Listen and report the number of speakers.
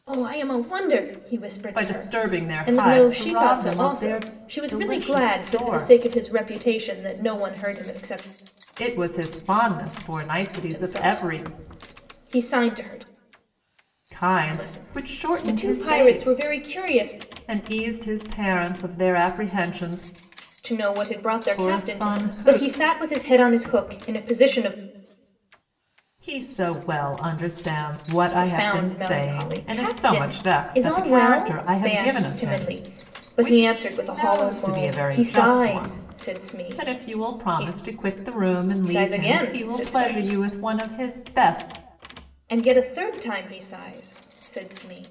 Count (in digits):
2